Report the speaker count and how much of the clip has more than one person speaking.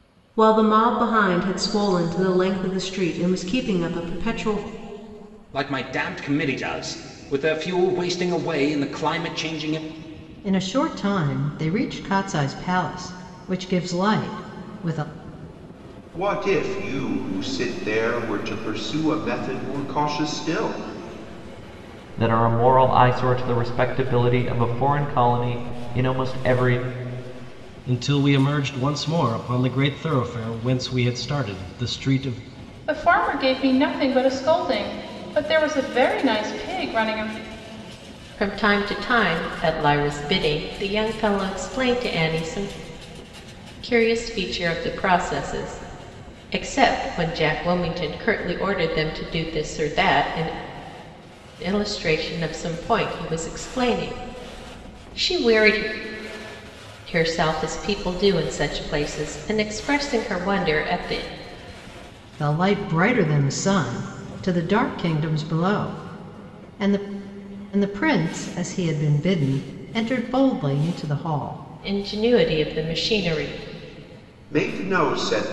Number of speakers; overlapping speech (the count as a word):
eight, no overlap